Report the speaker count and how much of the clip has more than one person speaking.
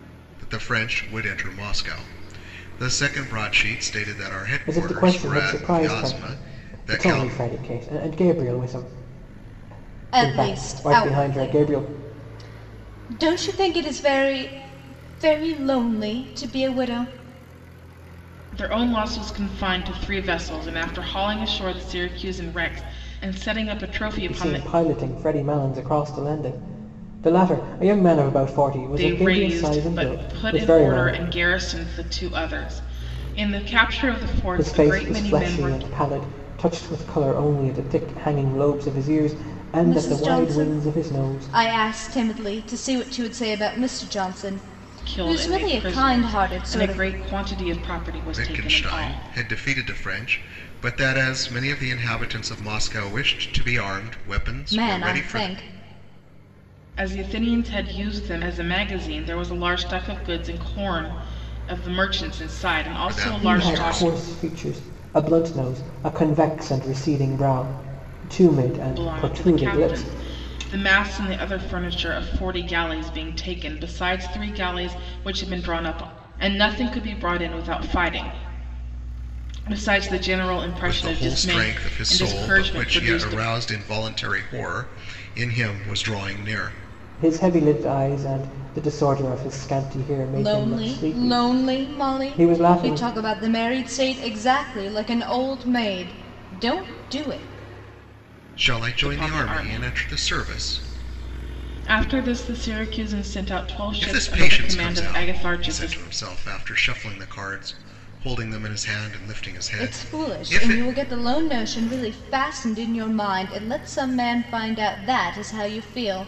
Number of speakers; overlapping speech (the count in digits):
4, about 23%